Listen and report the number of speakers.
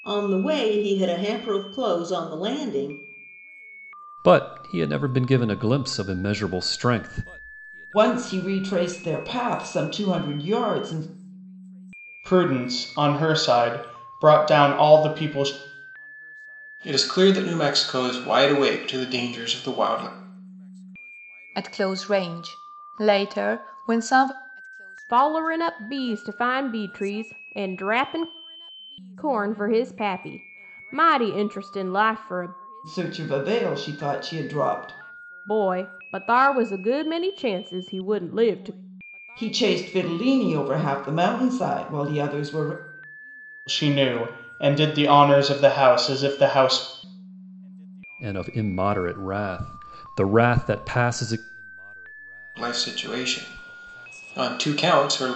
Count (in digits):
7